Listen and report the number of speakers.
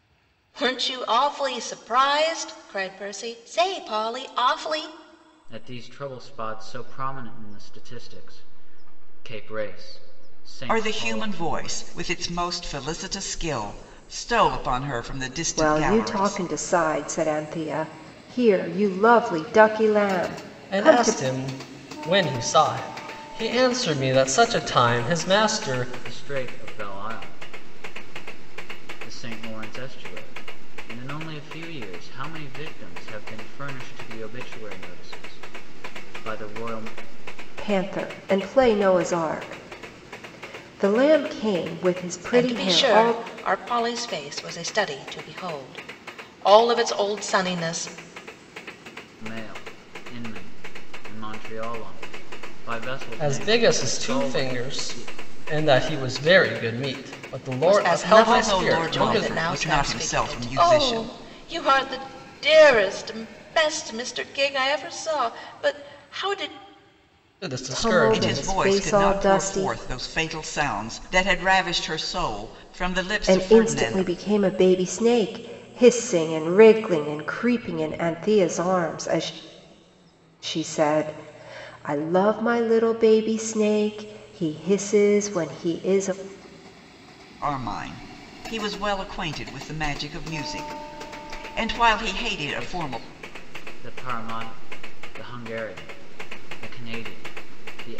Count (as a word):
five